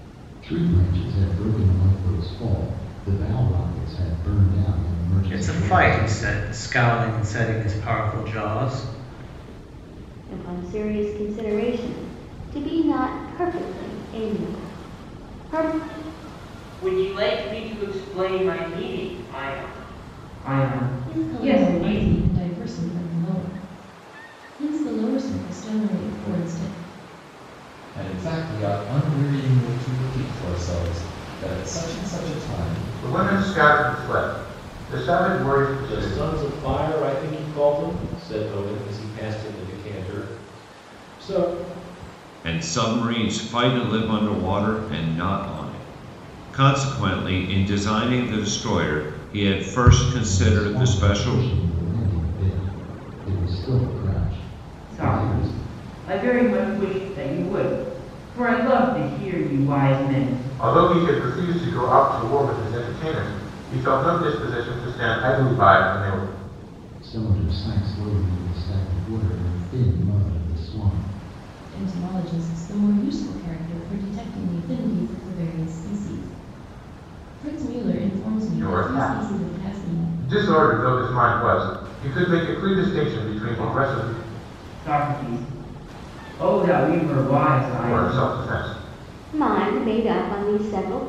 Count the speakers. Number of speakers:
nine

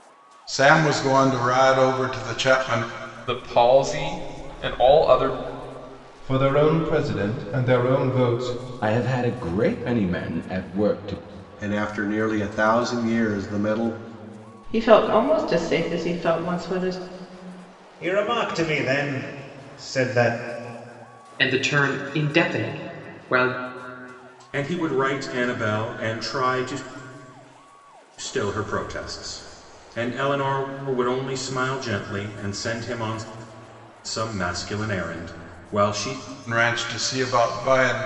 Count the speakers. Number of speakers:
nine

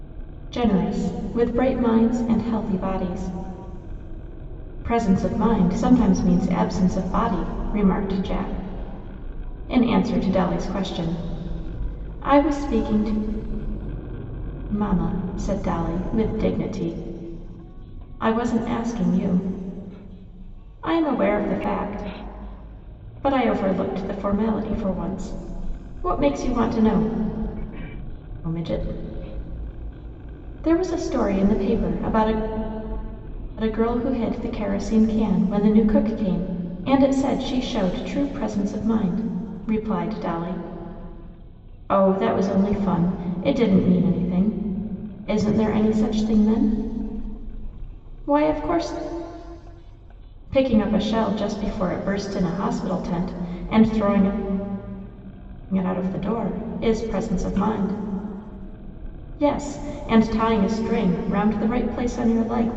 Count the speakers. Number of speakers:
one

